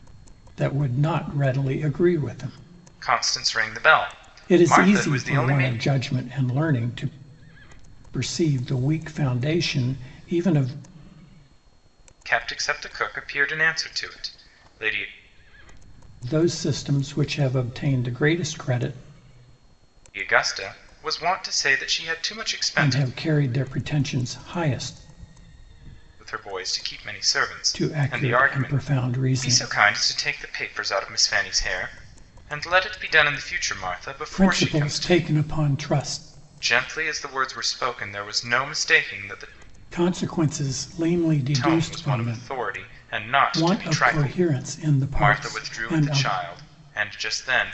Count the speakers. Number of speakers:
2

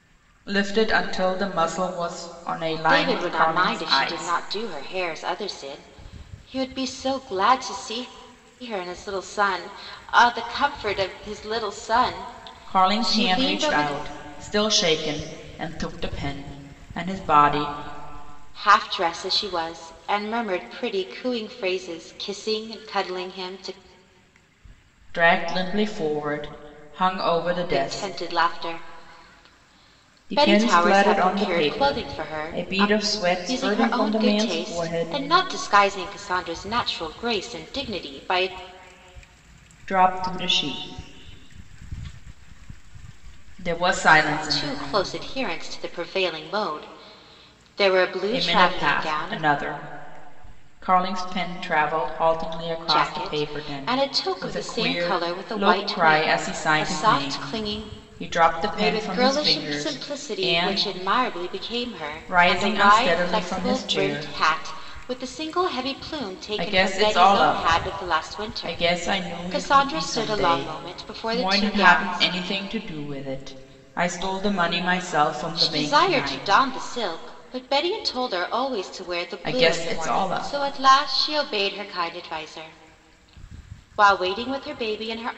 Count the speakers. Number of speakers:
2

